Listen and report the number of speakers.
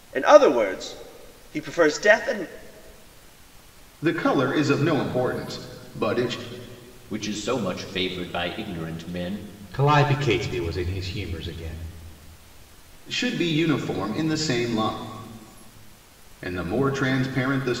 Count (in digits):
4